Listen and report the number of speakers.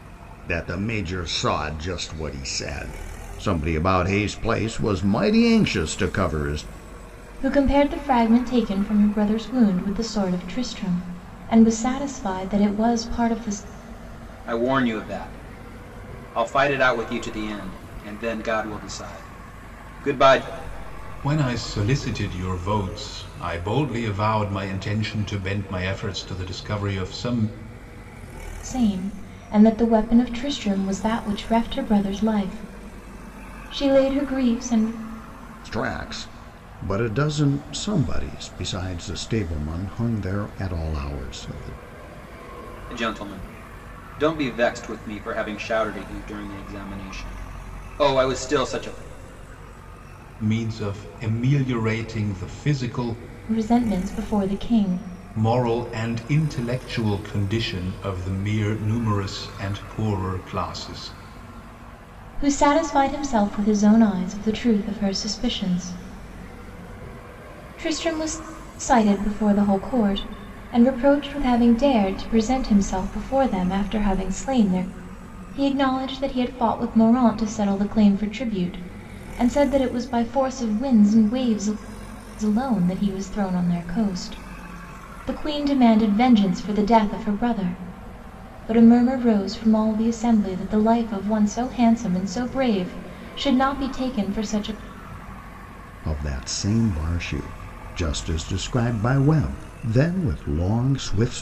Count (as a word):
four